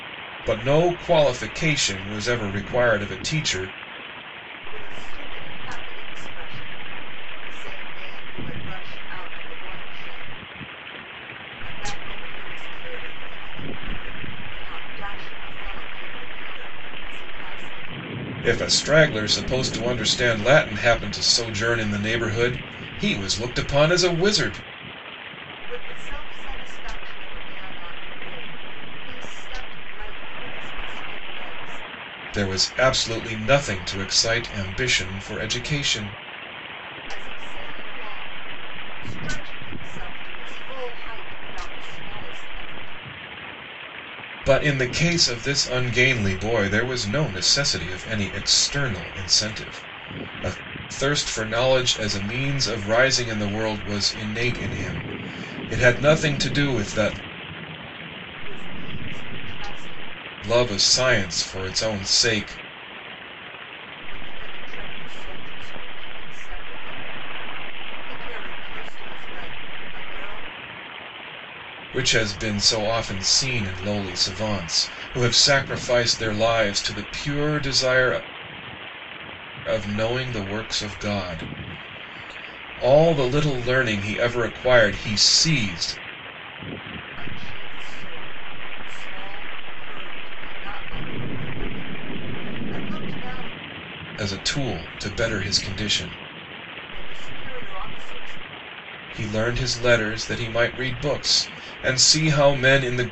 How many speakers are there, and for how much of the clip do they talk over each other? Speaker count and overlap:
two, no overlap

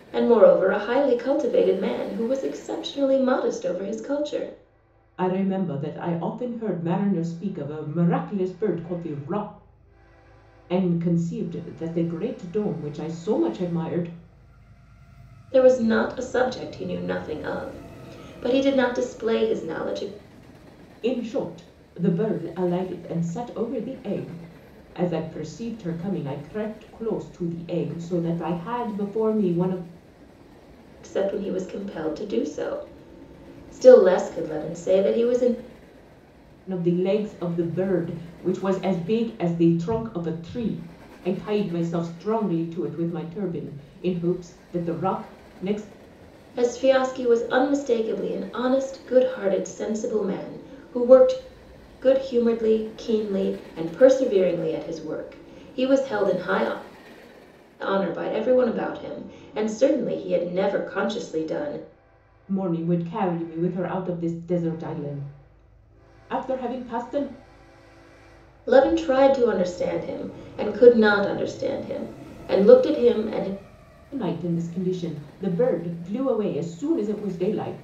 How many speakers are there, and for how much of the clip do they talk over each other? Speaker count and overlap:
two, no overlap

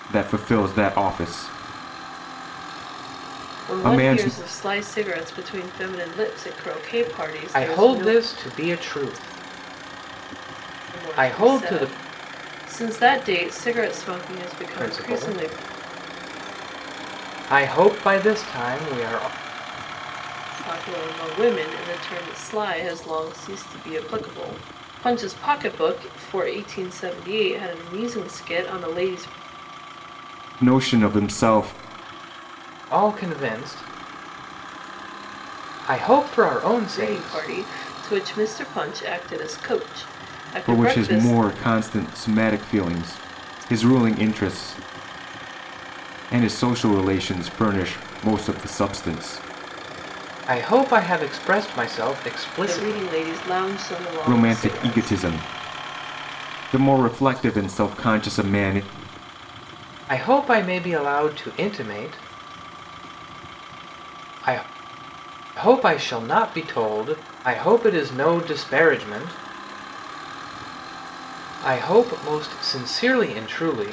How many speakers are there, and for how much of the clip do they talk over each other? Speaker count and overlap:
three, about 8%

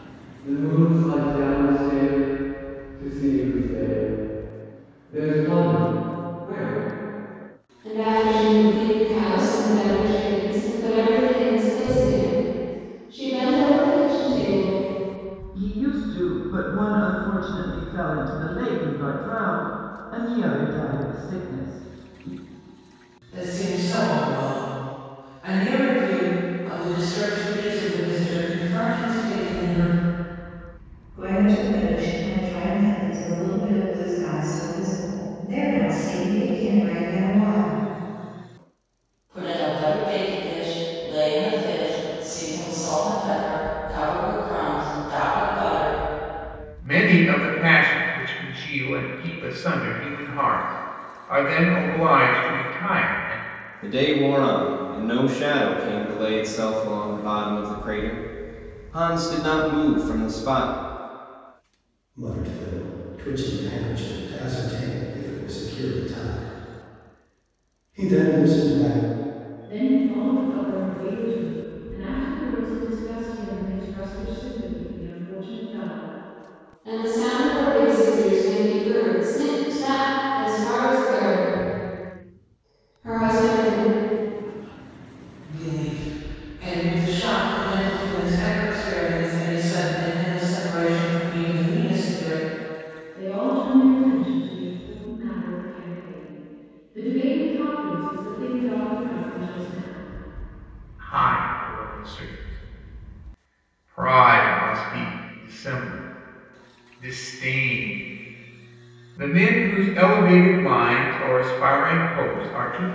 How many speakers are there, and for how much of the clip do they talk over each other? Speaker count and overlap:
ten, no overlap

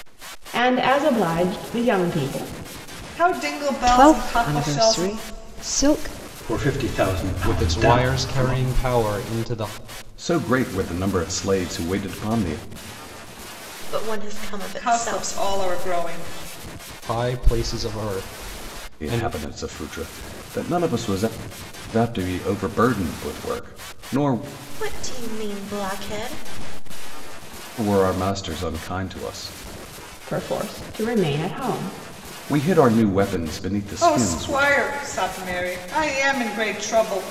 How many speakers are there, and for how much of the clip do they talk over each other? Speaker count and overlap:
seven, about 12%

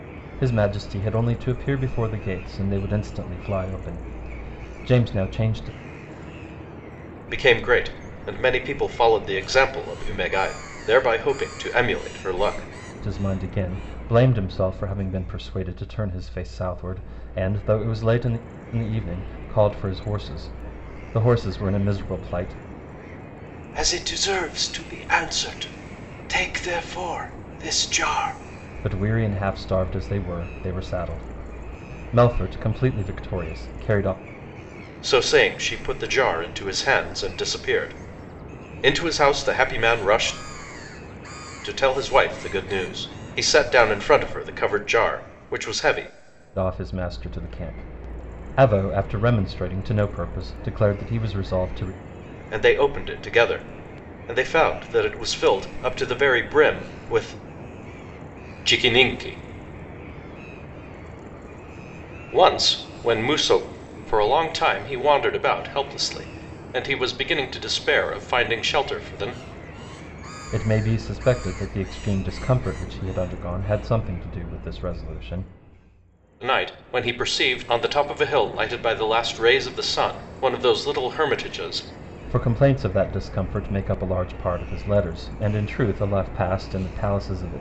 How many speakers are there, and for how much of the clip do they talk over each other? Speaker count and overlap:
two, no overlap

